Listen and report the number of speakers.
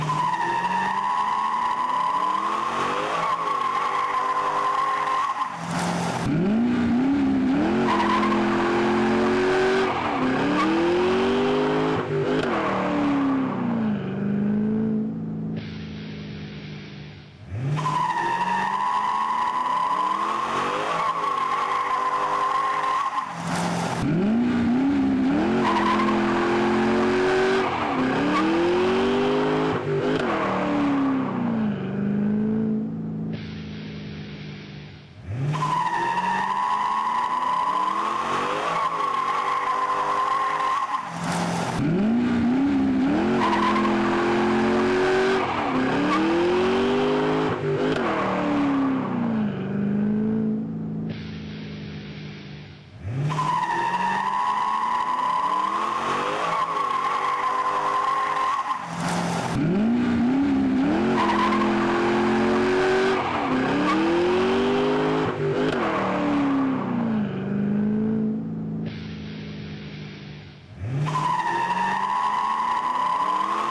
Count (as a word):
zero